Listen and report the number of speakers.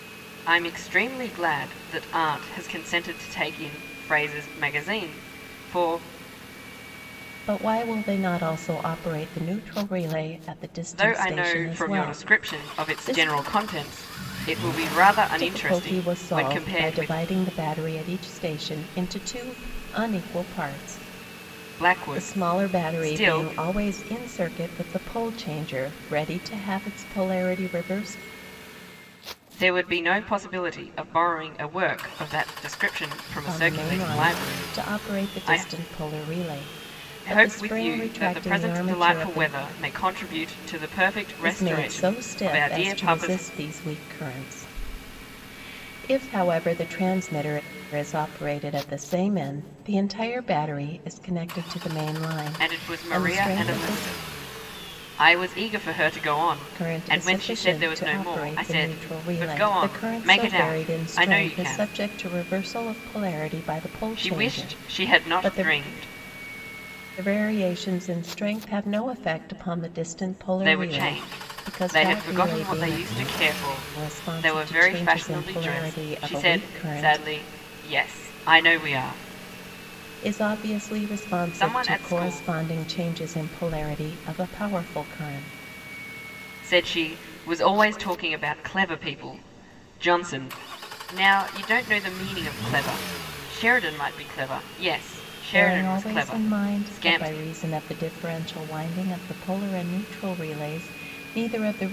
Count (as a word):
two